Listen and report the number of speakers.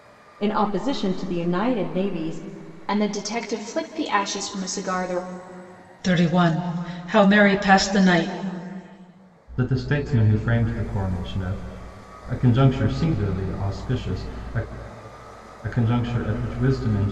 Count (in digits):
4